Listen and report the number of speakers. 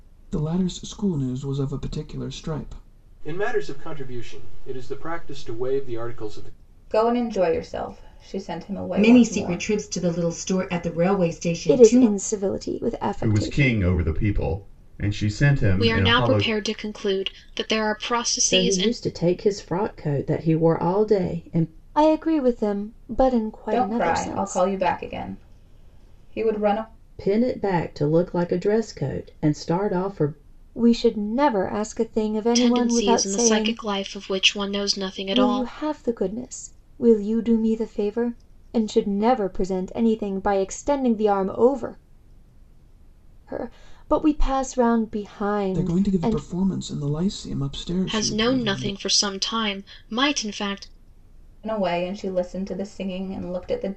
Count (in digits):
8